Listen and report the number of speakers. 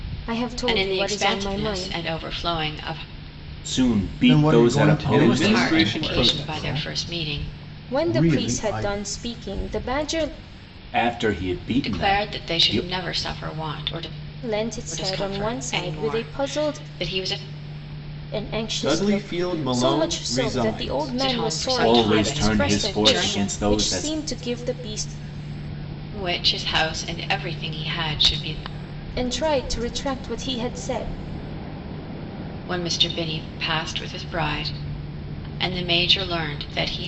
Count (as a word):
five